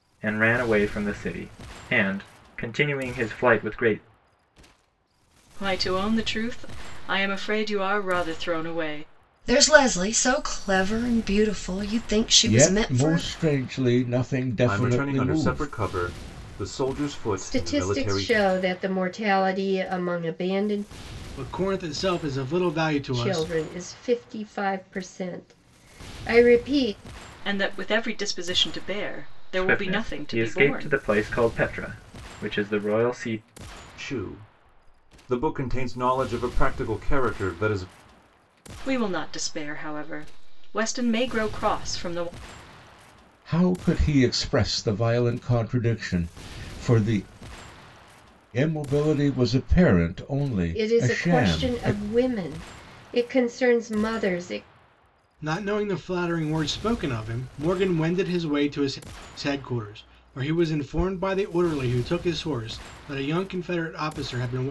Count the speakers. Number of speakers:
7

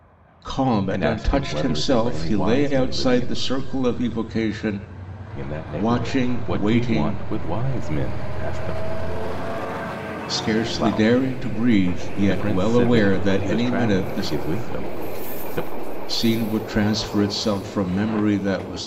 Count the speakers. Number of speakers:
2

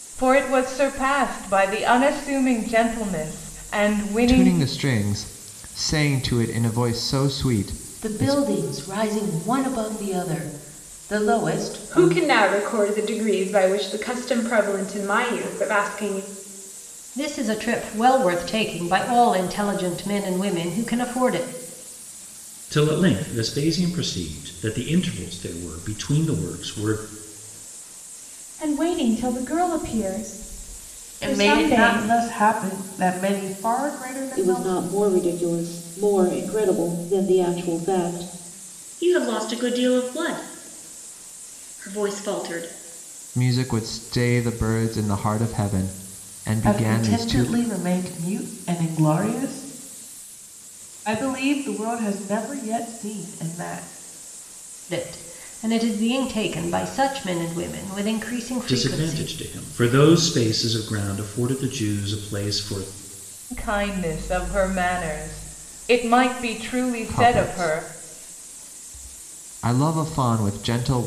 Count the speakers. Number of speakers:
10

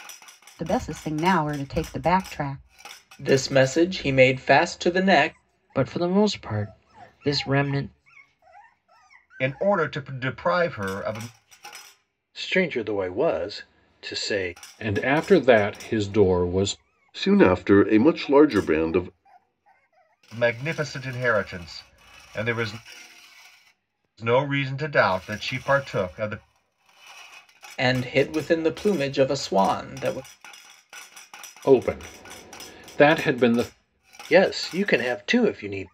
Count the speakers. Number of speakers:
7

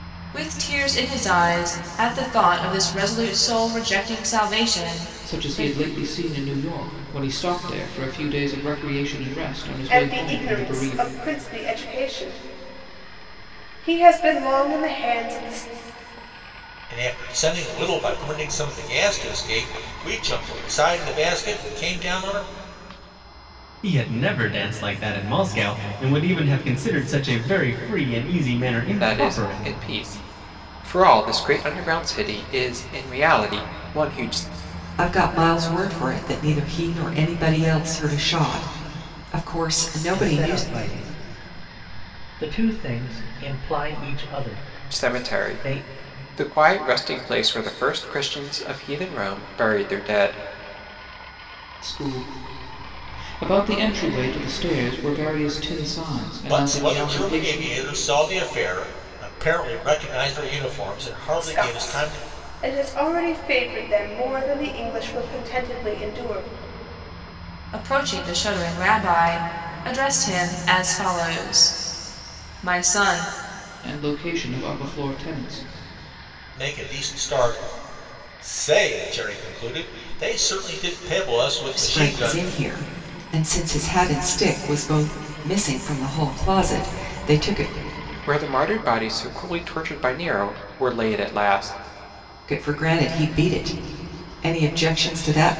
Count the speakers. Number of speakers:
8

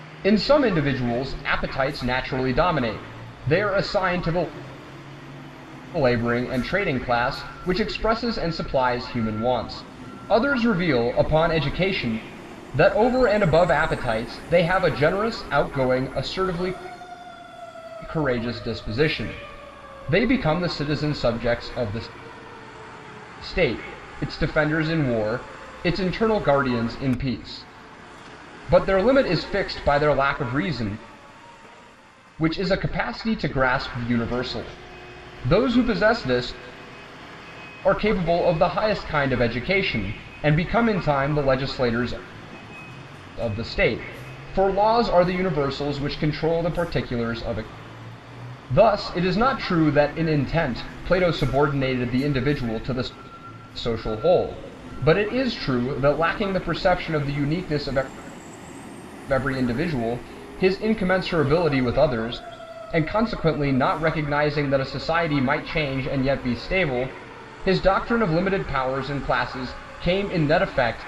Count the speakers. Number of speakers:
1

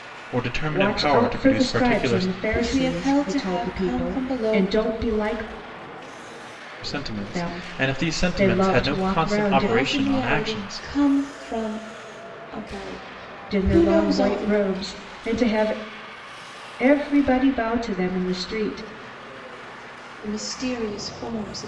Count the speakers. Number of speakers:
3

